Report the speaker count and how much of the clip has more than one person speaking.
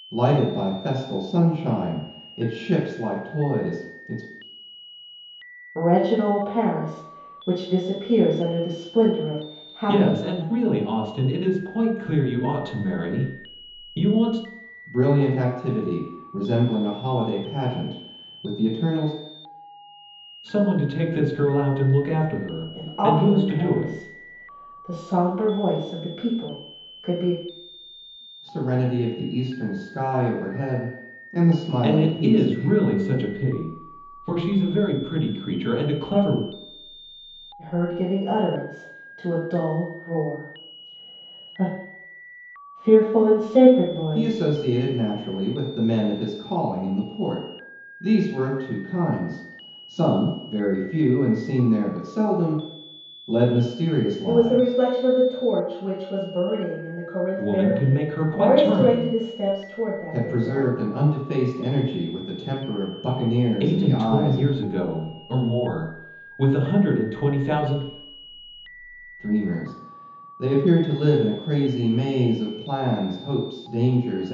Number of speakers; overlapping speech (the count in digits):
3, about 10%